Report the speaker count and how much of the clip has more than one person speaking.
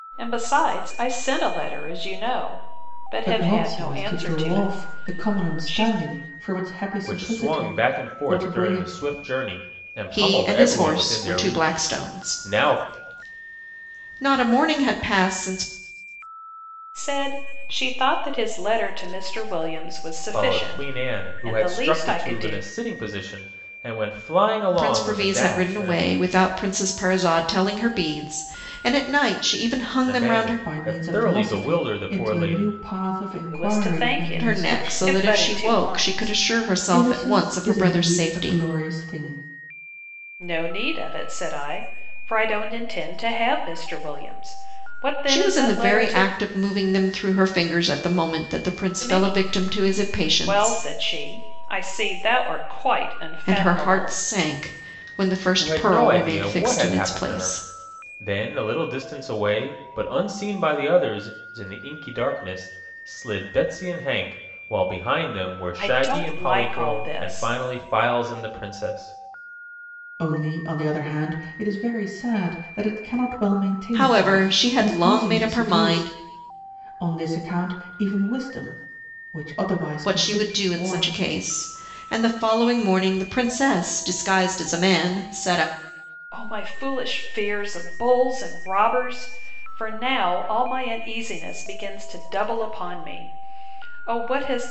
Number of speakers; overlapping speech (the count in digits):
4, about 31%